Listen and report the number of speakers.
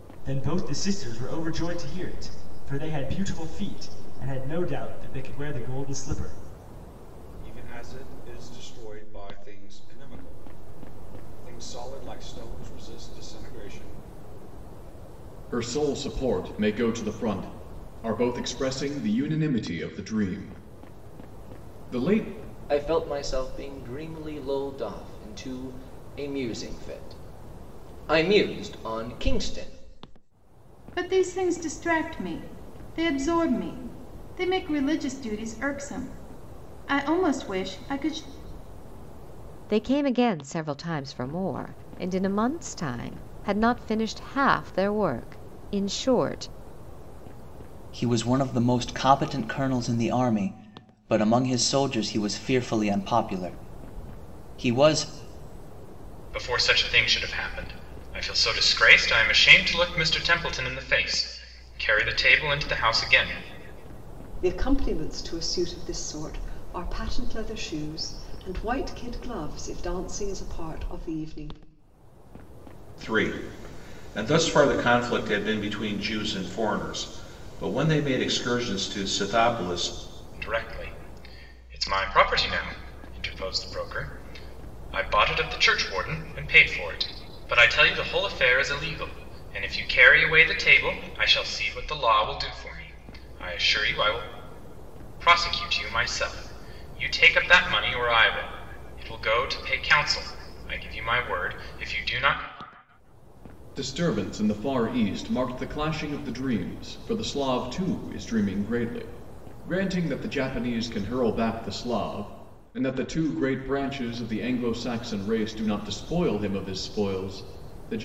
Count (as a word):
ten